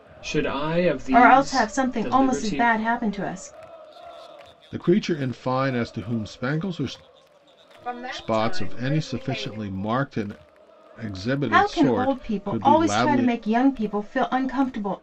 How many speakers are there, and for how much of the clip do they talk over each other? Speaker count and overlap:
4, about 33%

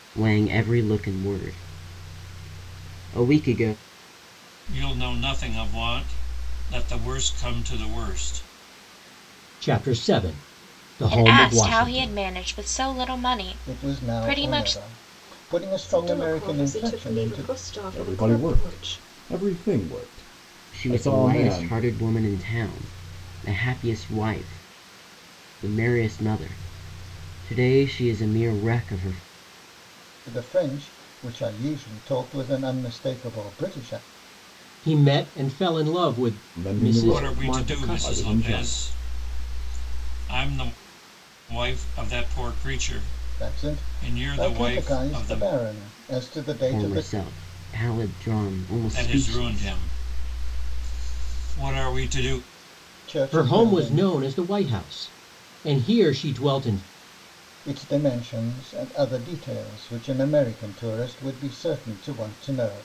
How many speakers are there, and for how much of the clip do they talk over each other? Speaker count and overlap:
7, about 20%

